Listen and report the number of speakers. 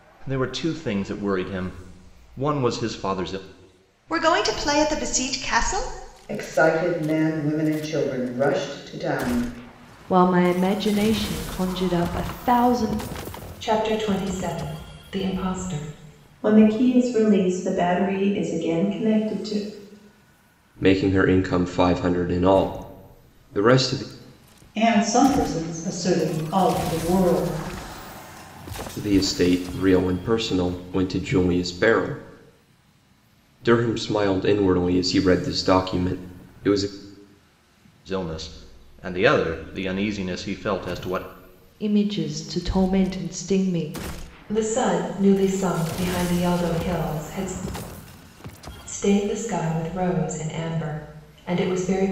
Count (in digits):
8